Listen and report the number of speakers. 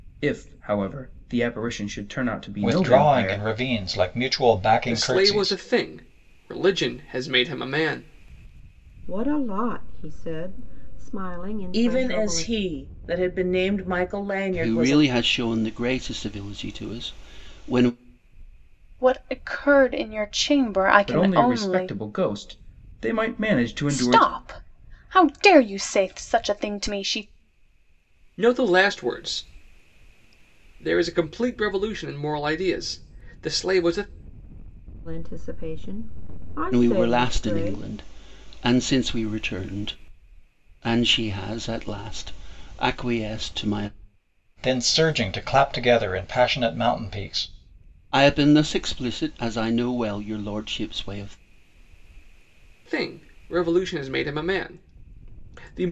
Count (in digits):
7